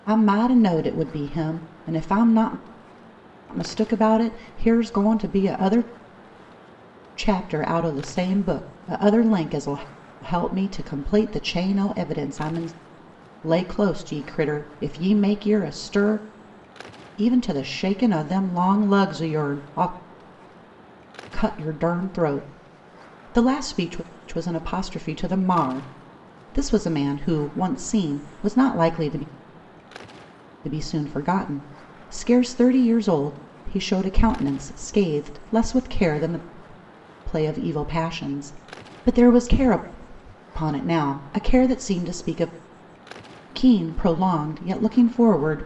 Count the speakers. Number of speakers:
1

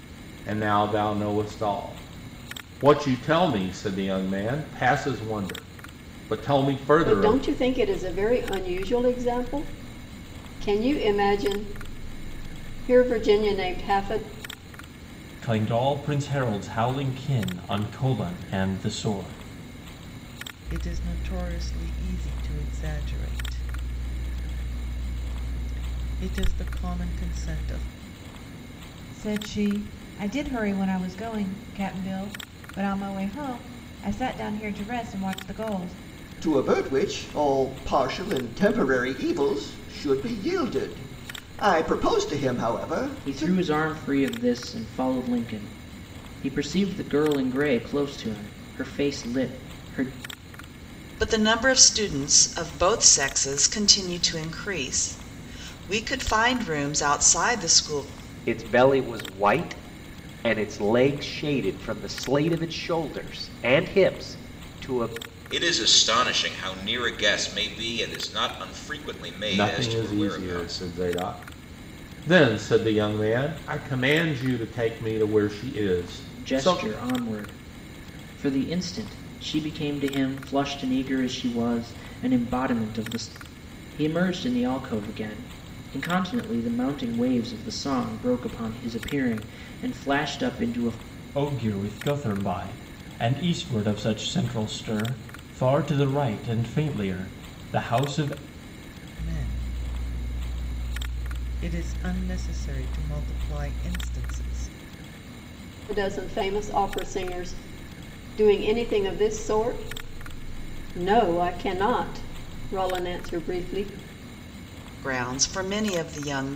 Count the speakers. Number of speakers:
10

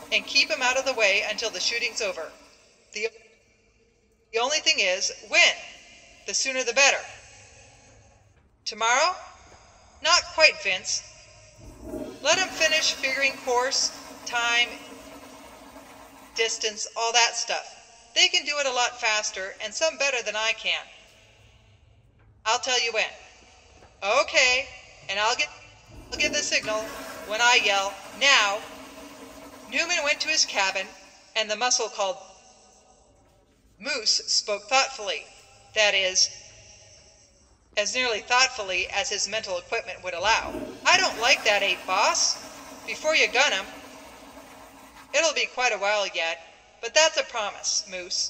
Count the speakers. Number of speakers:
1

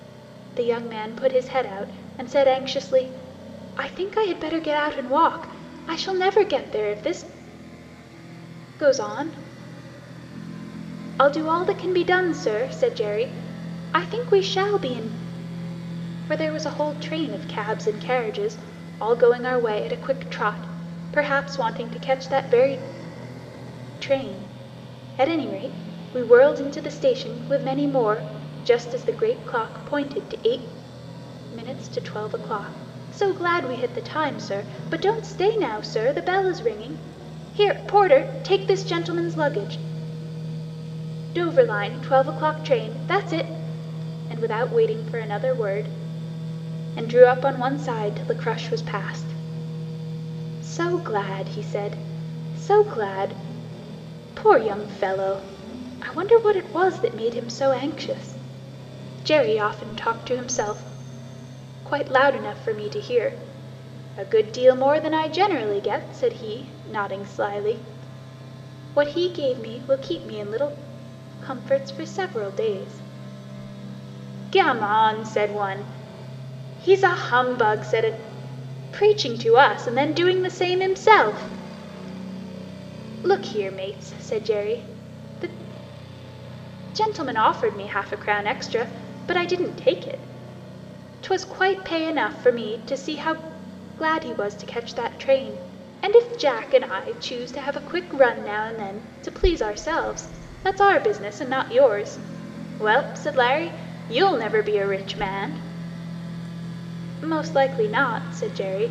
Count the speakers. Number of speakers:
1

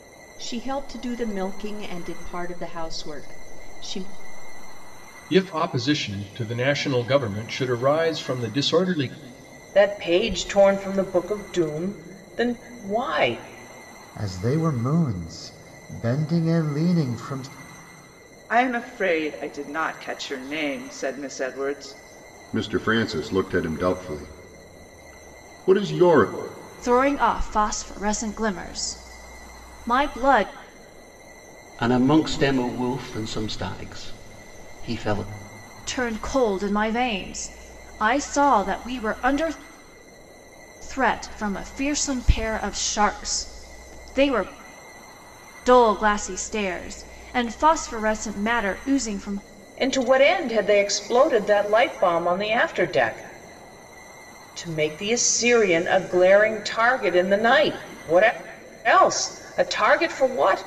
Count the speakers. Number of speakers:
8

